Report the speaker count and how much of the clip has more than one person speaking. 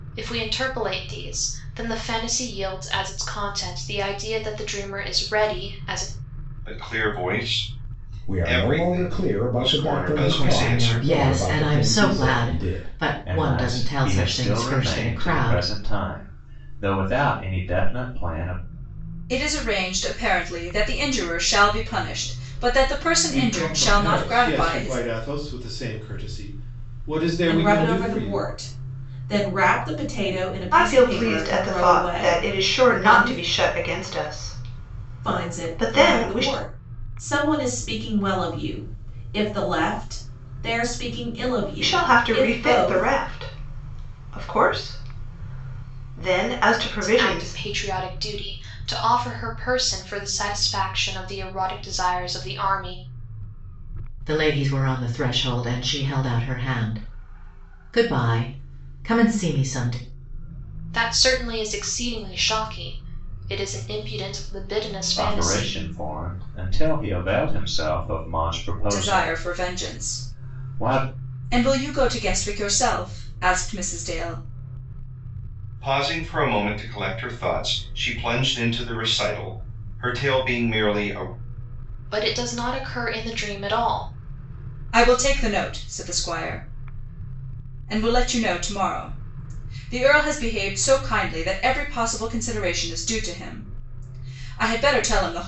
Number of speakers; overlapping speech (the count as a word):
nine, about 20%